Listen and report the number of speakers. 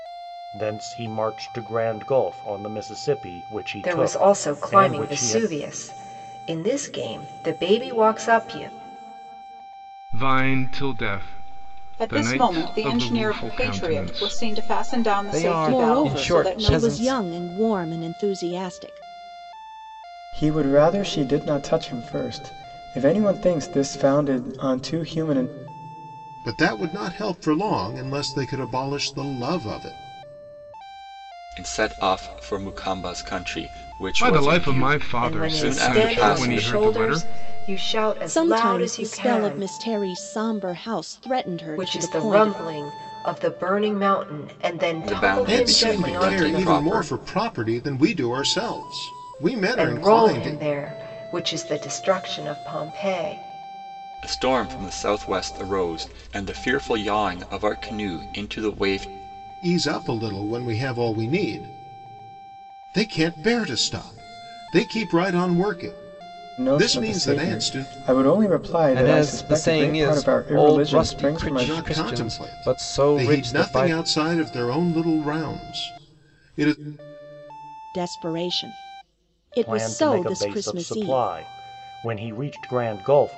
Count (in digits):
9